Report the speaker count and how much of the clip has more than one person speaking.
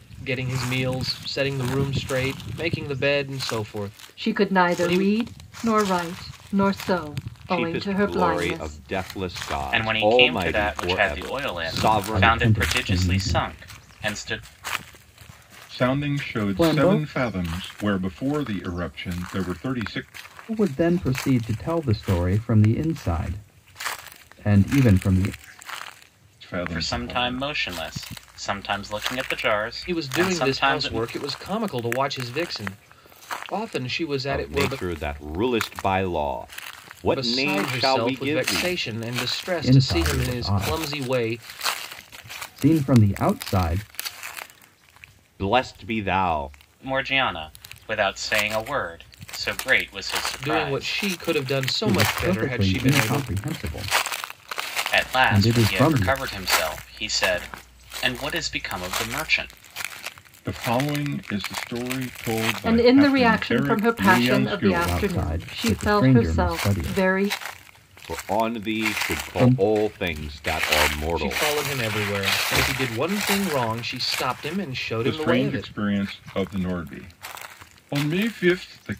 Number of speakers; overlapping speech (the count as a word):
six, about 34%